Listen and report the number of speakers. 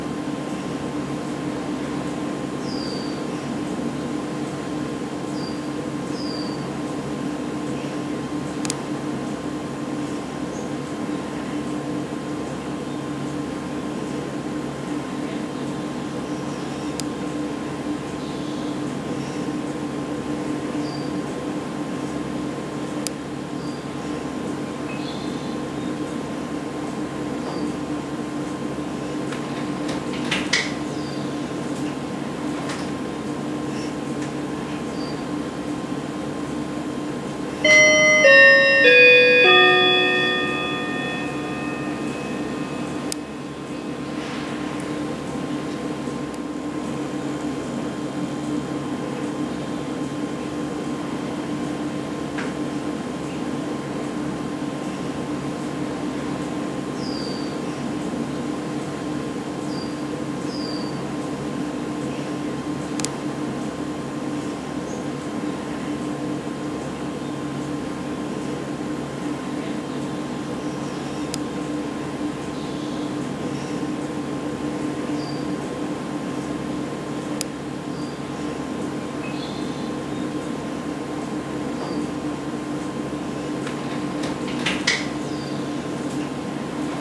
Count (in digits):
0